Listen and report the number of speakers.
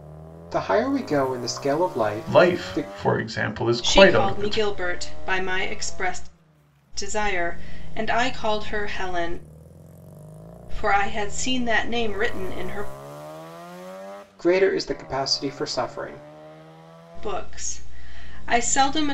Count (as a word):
three